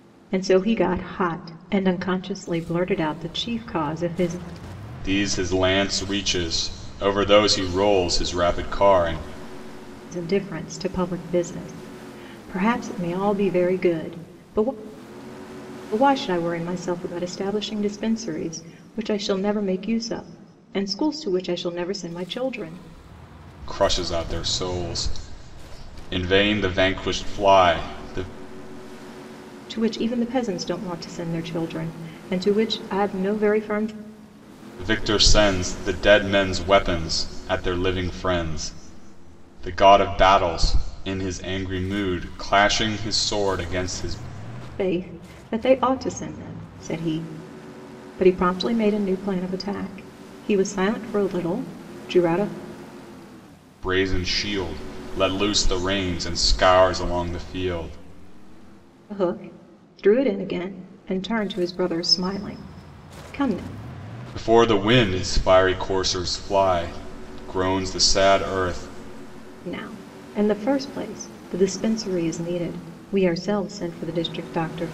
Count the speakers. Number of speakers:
two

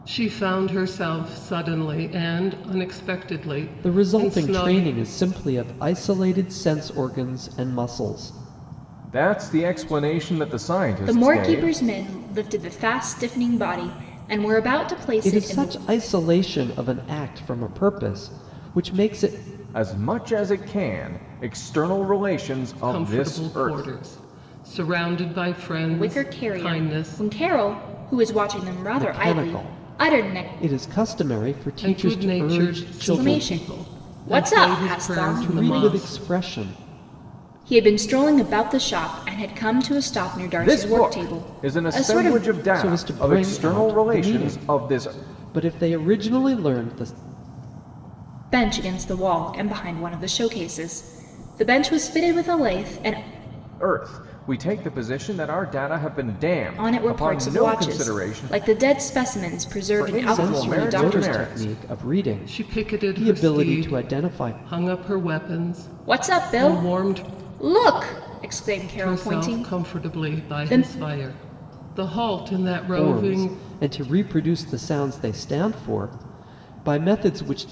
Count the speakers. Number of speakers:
four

